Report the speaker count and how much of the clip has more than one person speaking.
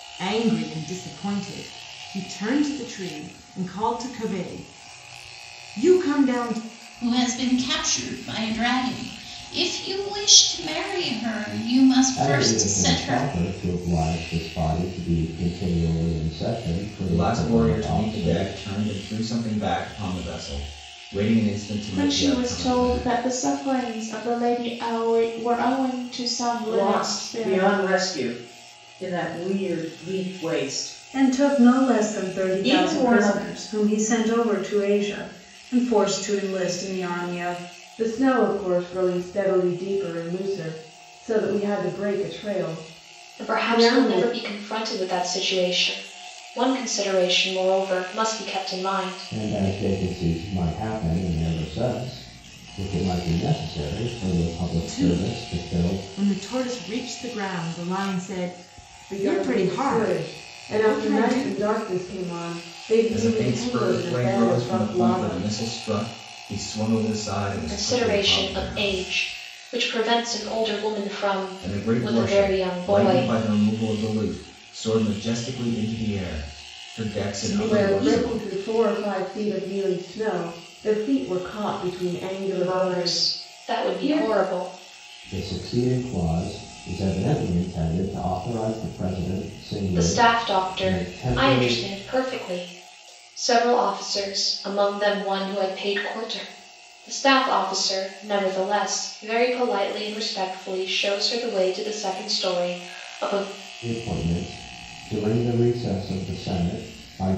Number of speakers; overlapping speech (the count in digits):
9, about 21%